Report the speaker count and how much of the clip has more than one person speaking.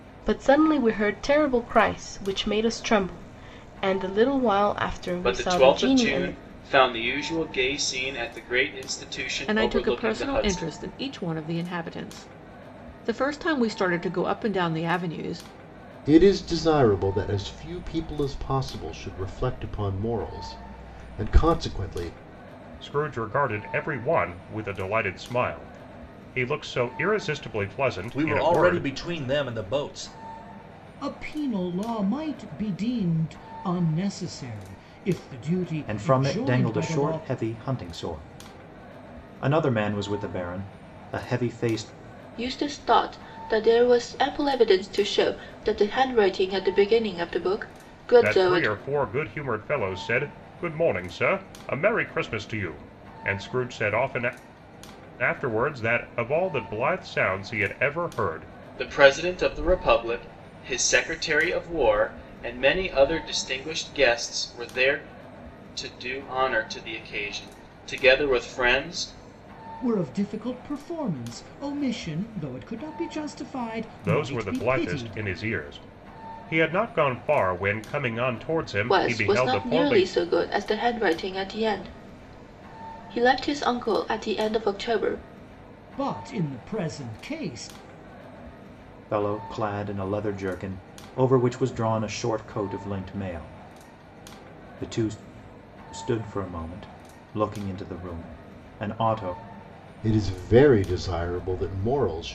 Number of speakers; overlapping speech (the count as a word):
nine, about 8%